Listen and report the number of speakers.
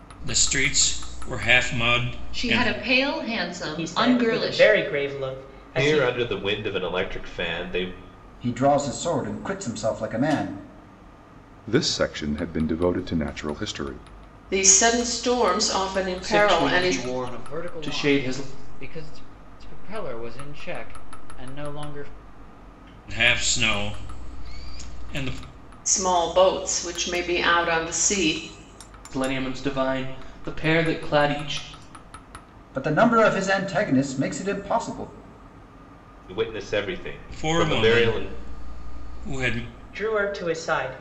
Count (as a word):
nine